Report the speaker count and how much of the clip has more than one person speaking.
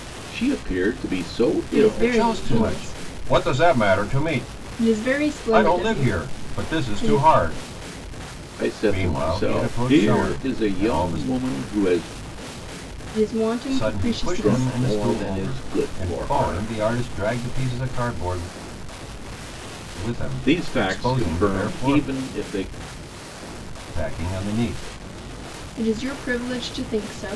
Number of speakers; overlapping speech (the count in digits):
3, about 37%